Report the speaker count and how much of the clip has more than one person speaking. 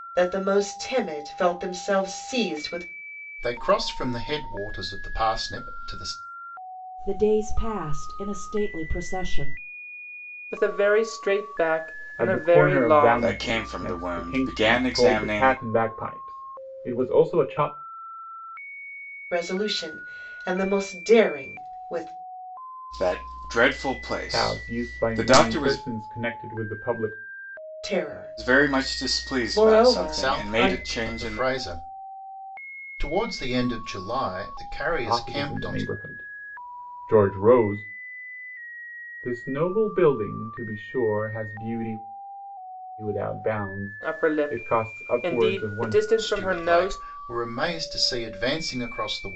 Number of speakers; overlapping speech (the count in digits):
6, about 24%